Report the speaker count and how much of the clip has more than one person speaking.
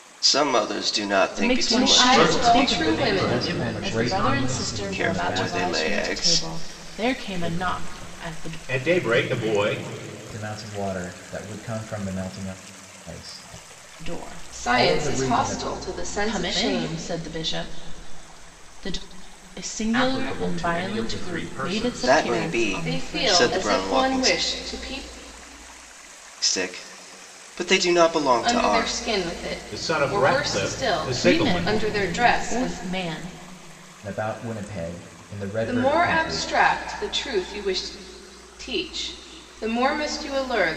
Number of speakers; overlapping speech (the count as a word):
six, about 45%